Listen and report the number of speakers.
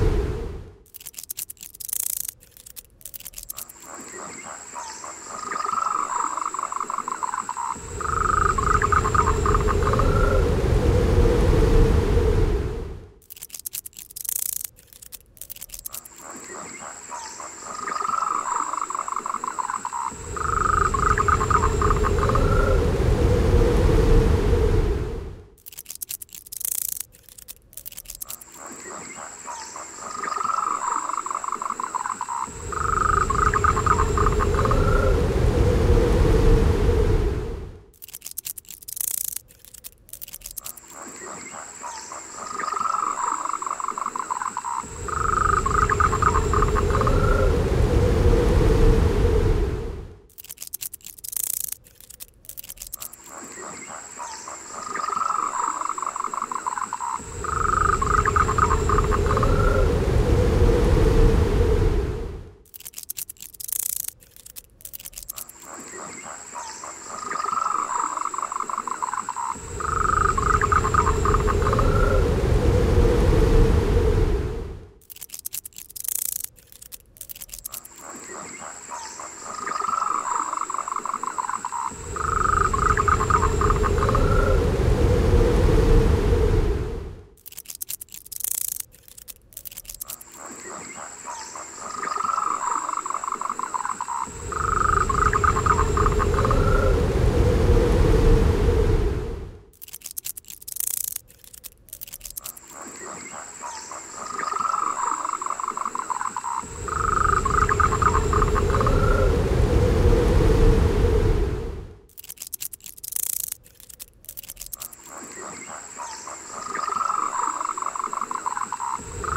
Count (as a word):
zero